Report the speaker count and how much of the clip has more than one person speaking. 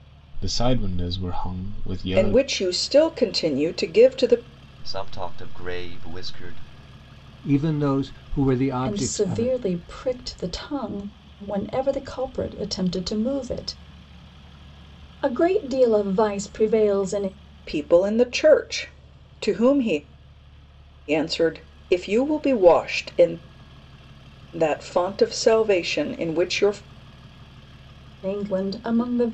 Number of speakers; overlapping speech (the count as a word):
five, about 4%